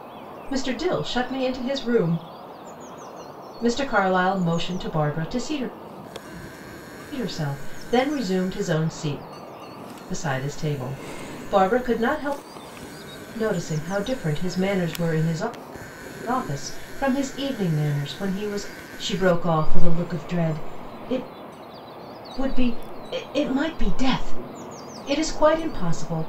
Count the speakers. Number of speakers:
one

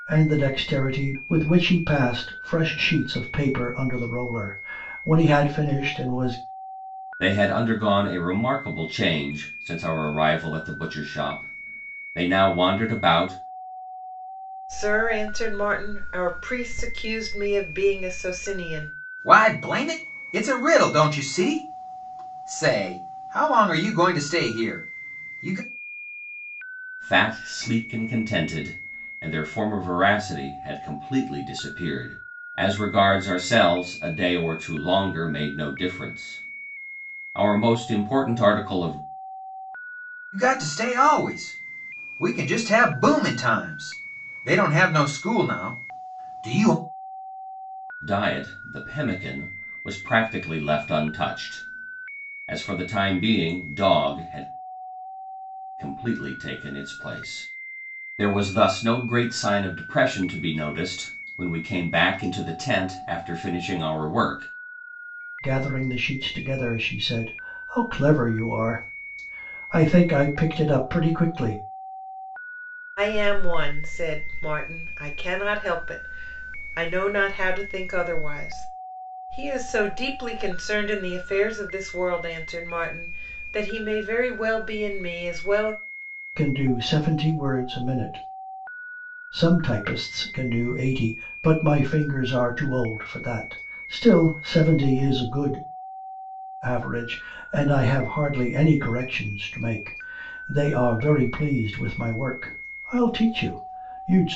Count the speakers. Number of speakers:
four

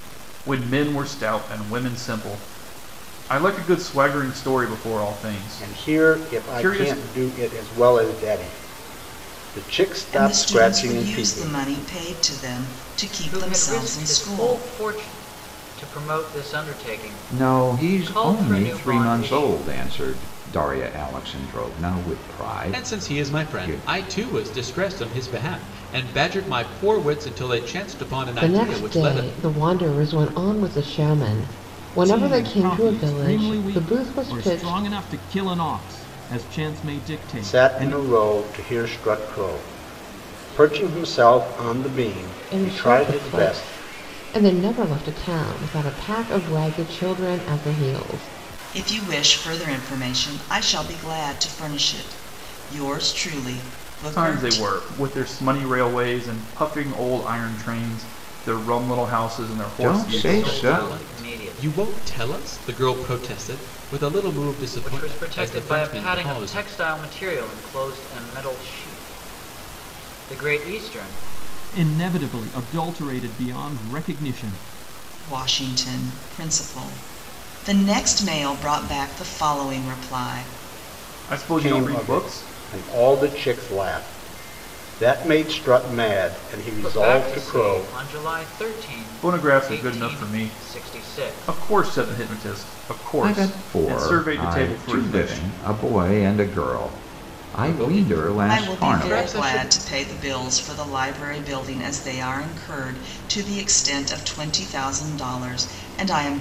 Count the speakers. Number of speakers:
eight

